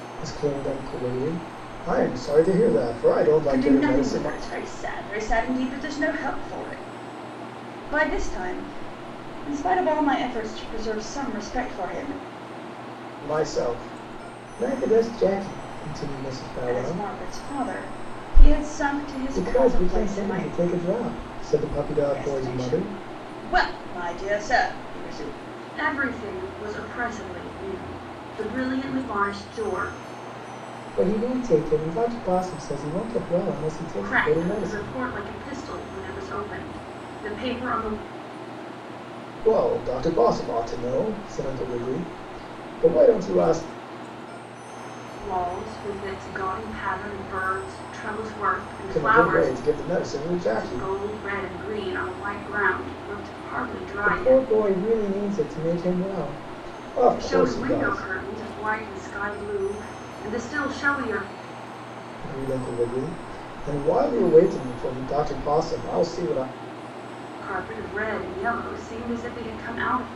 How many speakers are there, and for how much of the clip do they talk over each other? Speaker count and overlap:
2, about 10%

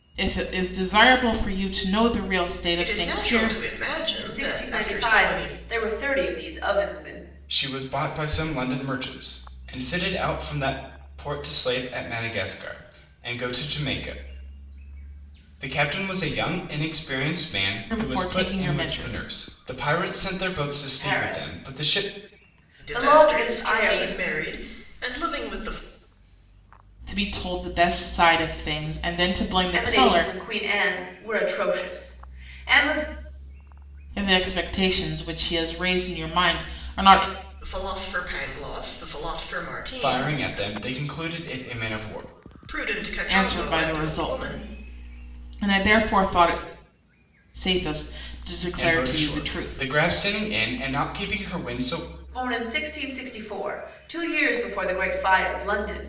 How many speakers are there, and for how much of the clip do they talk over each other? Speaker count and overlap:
4, about 18%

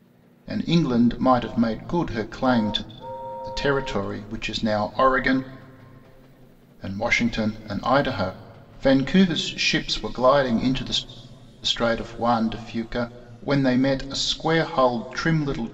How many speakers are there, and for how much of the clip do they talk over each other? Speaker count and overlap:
1, no overlap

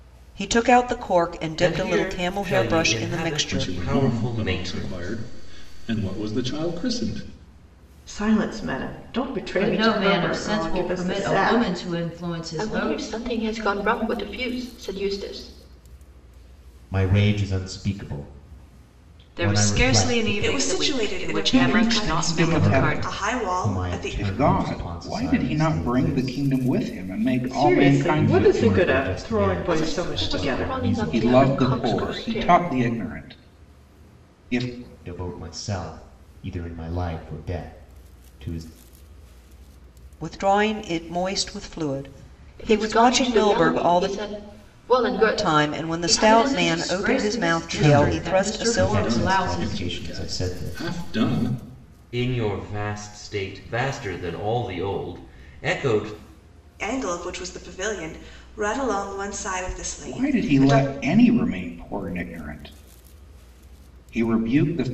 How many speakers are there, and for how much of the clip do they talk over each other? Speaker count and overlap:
10, about 41%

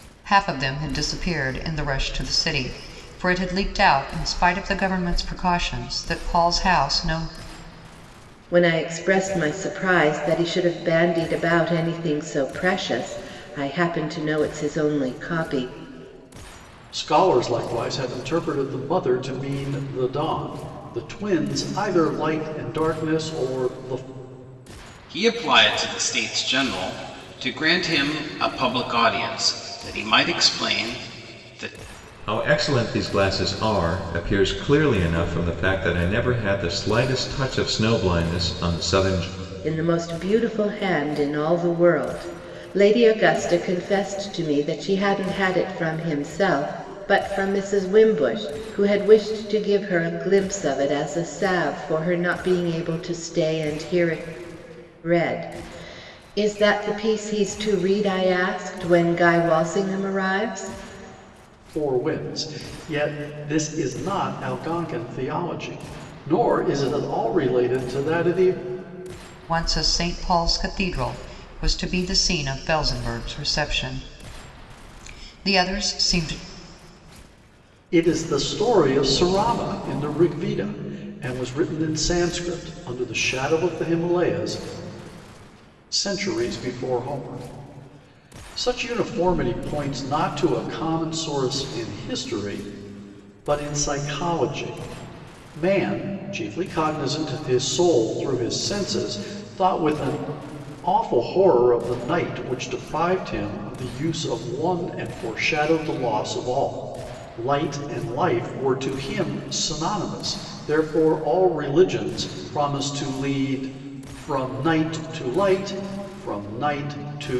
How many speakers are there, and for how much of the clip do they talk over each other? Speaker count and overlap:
5, no overlap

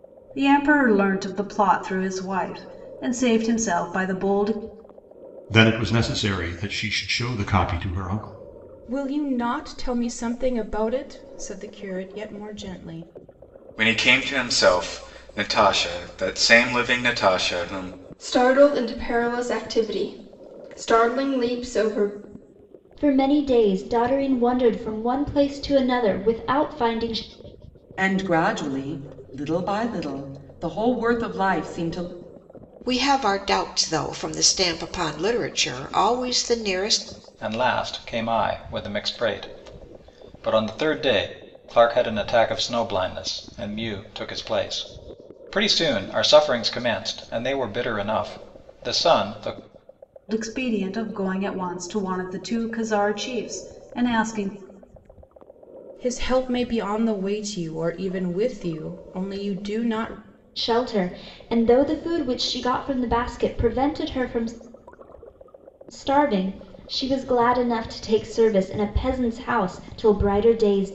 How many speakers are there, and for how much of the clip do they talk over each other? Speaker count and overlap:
9, no overlap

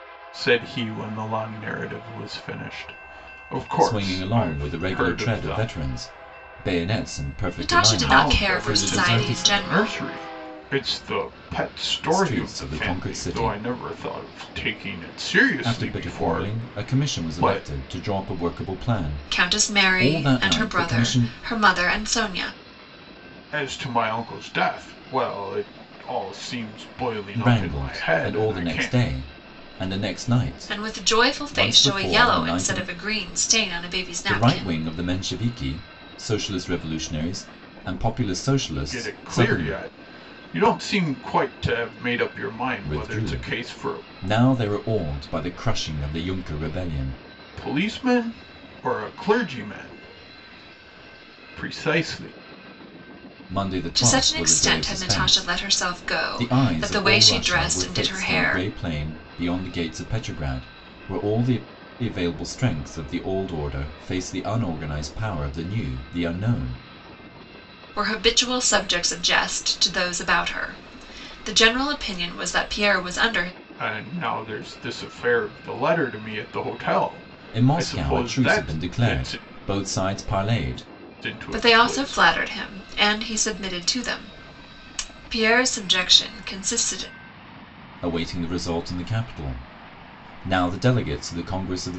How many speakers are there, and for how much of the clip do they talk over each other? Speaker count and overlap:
3, about 25%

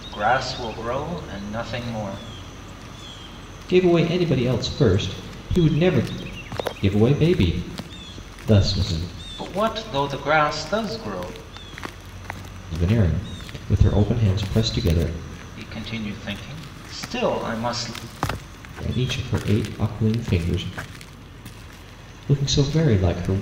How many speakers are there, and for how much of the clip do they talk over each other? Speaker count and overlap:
2, no overlap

